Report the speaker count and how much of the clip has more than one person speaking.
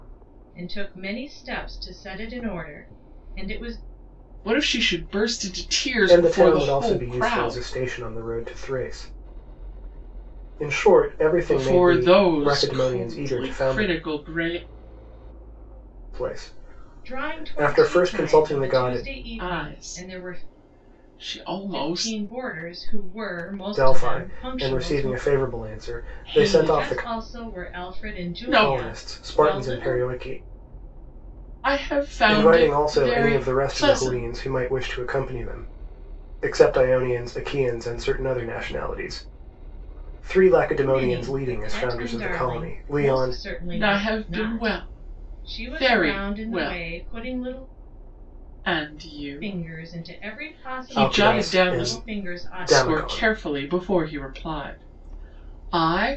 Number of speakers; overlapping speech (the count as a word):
three, about 45%